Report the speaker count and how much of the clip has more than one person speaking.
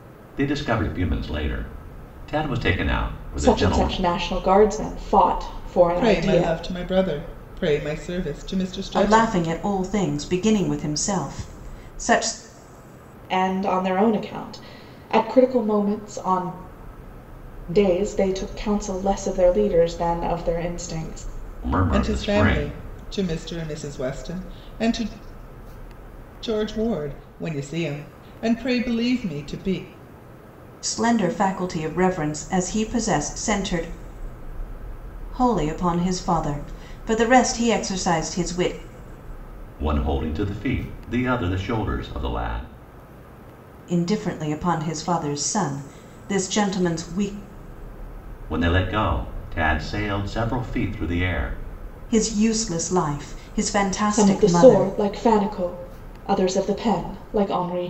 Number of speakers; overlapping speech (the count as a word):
four, about 6%